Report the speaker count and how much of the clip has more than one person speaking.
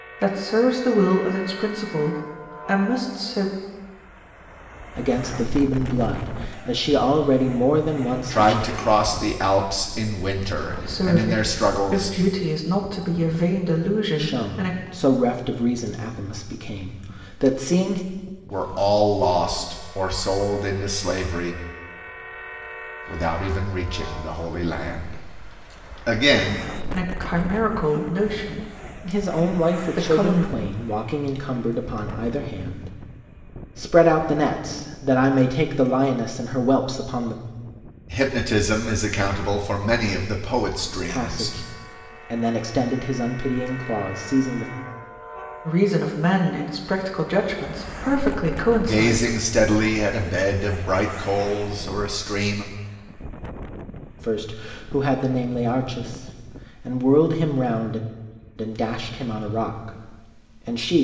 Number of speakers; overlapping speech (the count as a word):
three, about 8%